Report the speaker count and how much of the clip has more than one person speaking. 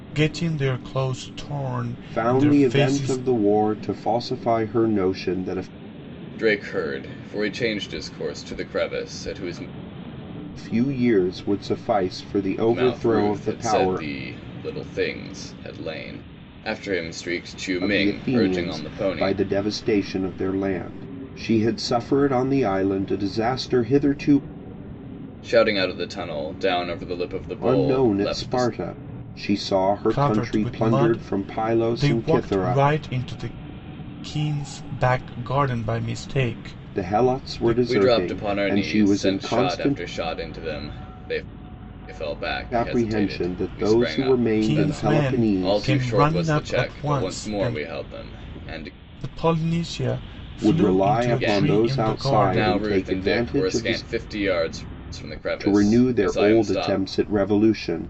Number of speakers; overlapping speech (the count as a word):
three, about 37%